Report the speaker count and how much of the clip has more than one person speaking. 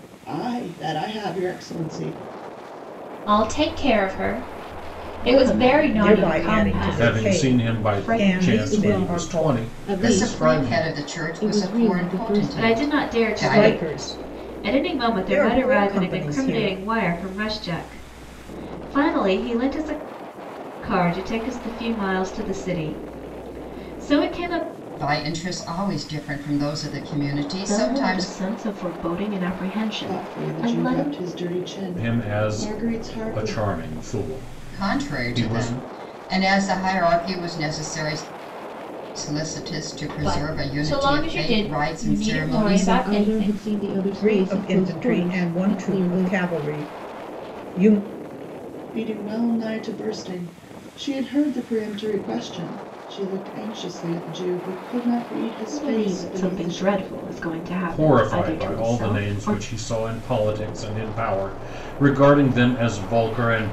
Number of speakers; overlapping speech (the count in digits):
8, about 39%